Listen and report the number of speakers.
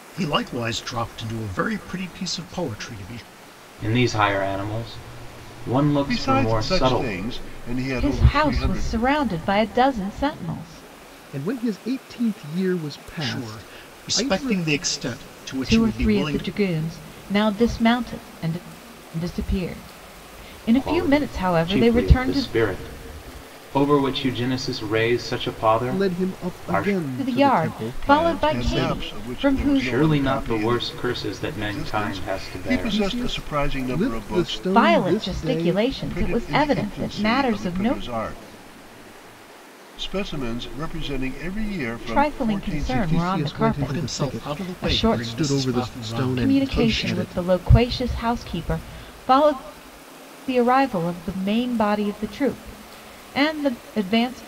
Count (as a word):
five